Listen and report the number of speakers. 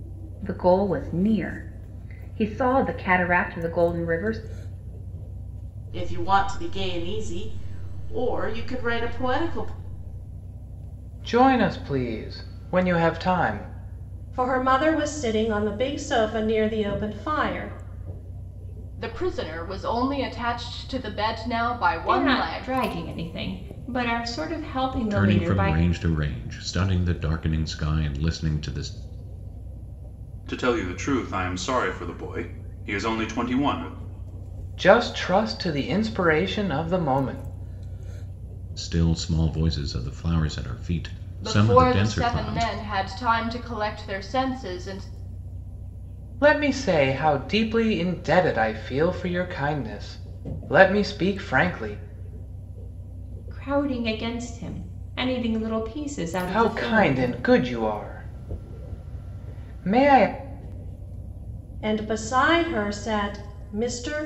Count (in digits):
8